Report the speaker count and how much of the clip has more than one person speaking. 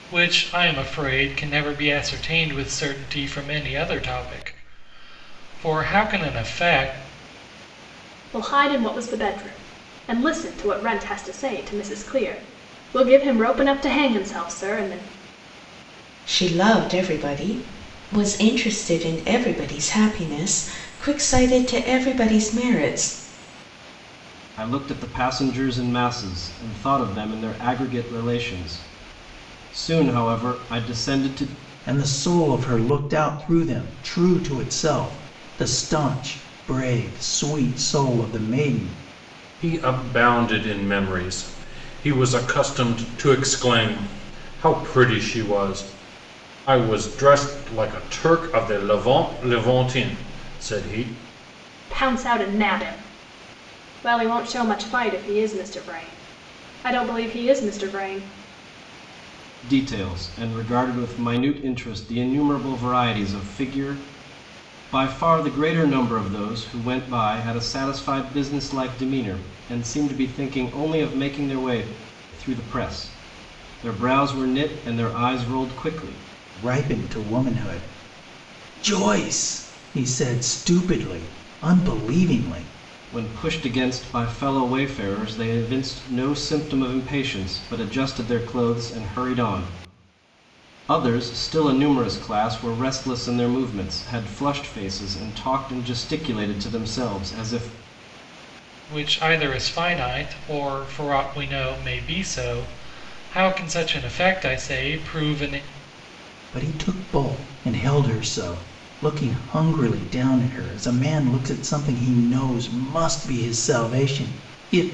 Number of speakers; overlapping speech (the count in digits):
6, no overlap